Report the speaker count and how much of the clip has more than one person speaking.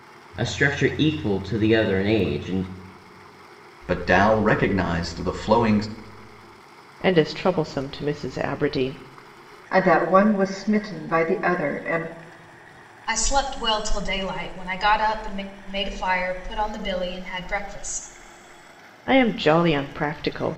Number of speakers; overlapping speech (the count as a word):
five, no overlap